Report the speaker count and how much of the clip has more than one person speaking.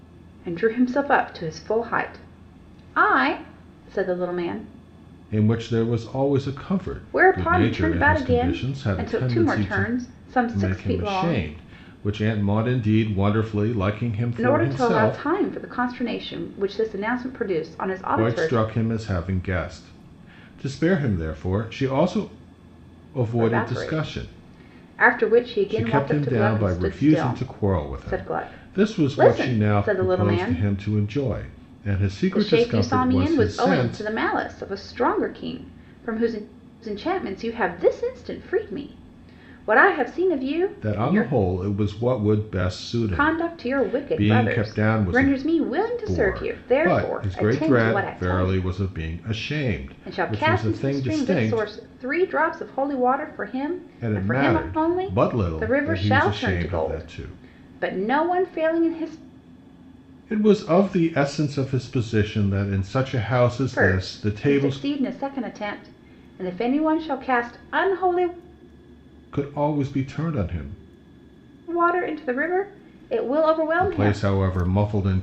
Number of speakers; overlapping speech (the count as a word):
two, about 33%